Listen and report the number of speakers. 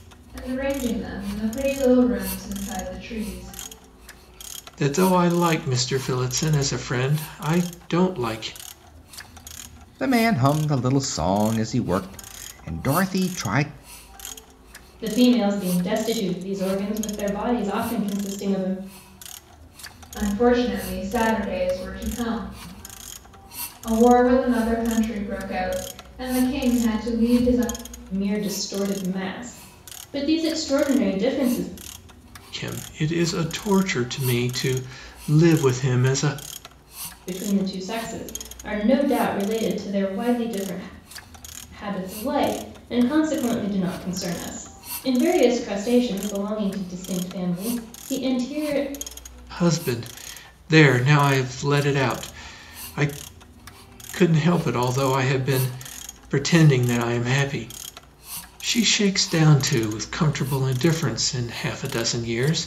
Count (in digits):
4